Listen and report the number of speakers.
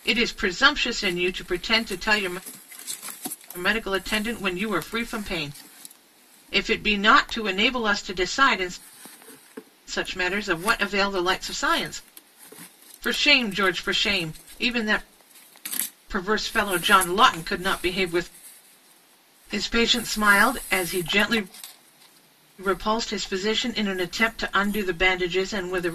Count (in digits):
1